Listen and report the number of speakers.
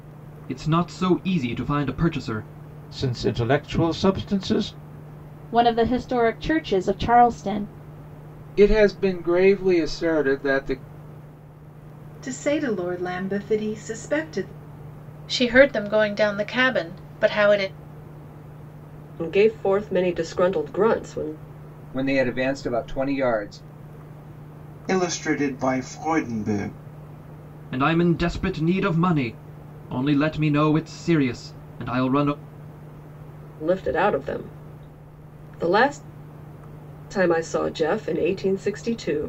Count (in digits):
9